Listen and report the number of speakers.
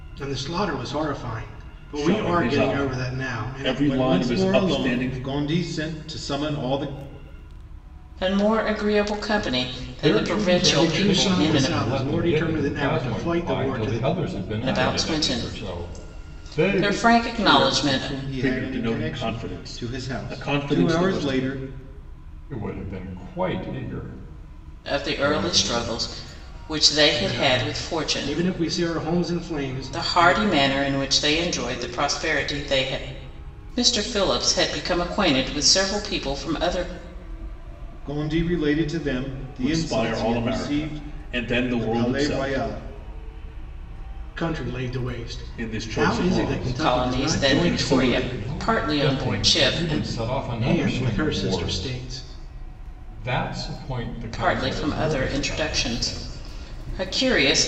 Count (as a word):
five